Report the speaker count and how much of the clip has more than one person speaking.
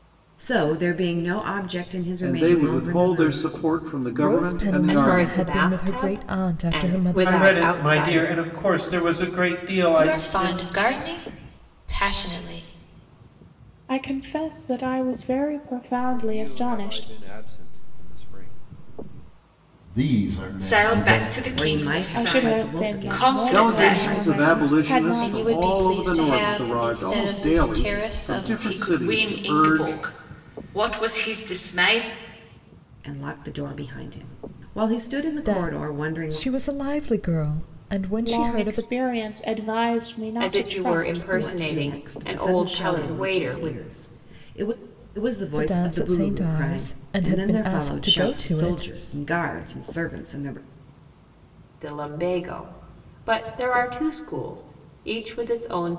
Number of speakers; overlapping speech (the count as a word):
ten, about 44%